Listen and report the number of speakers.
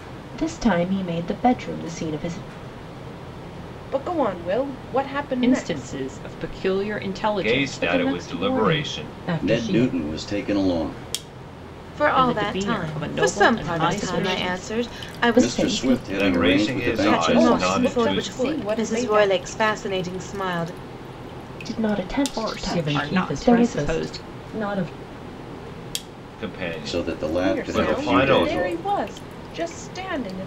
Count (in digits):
7